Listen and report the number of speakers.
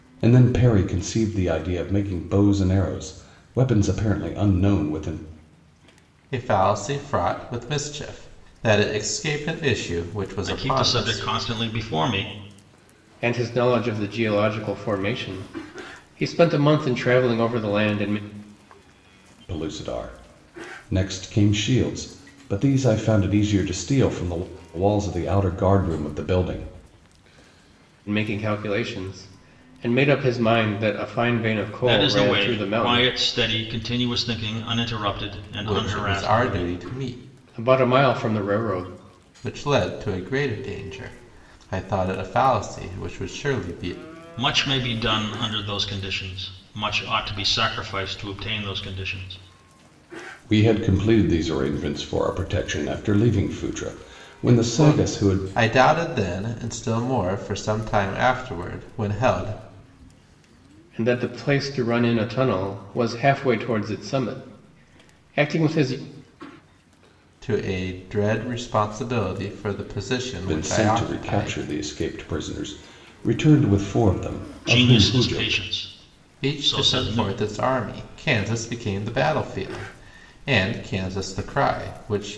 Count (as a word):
four